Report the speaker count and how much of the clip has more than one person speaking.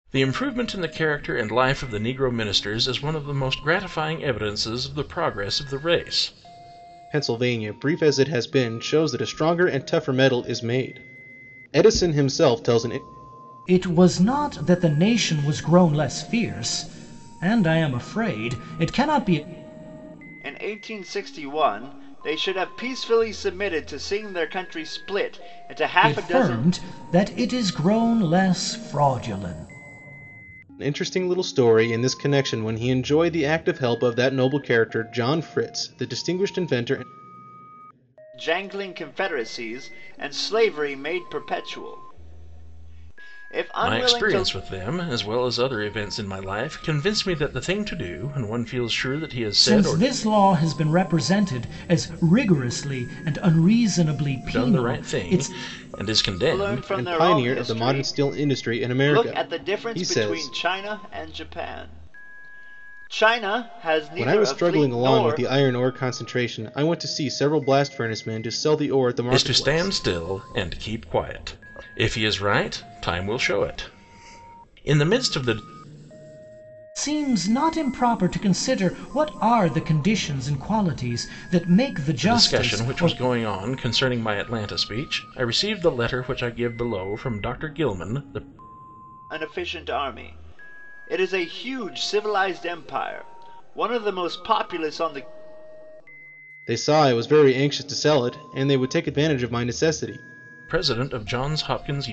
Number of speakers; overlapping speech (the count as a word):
four, about 9%